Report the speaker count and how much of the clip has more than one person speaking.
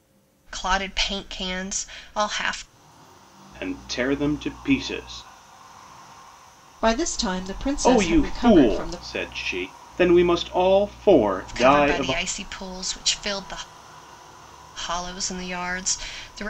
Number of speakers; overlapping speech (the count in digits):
3, about 12%